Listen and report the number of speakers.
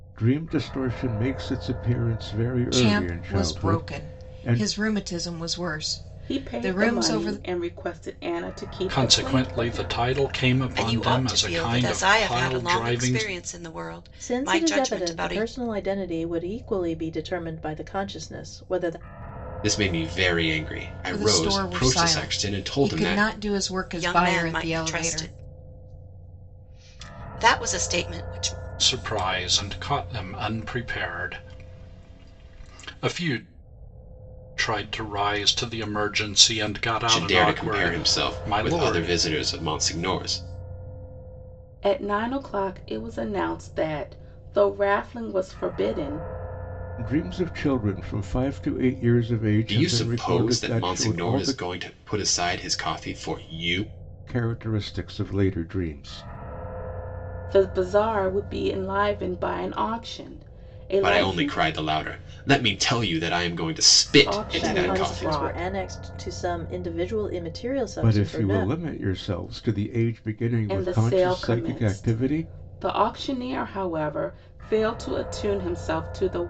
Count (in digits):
7